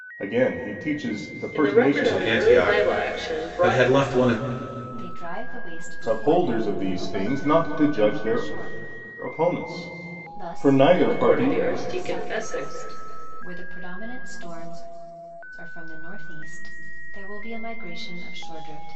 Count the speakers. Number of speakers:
4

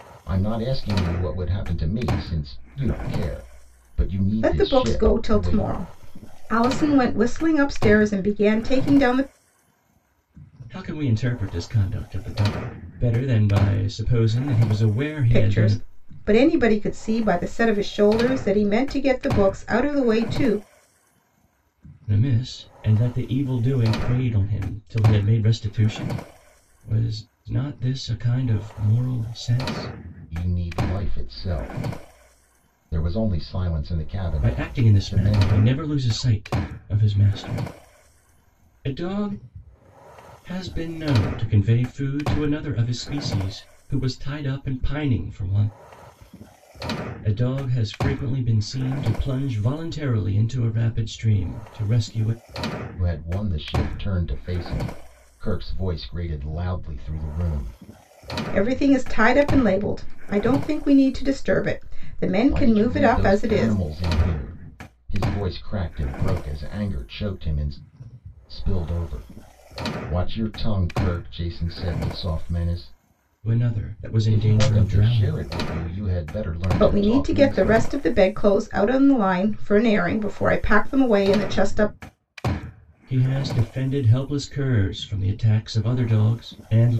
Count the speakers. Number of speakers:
3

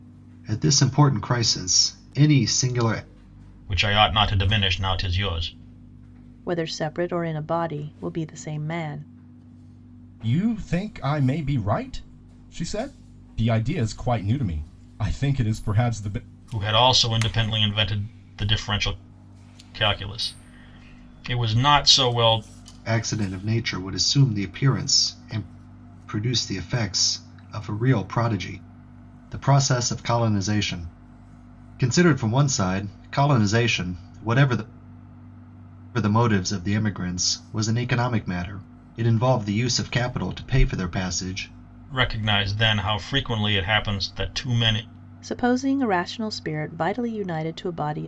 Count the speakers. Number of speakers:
4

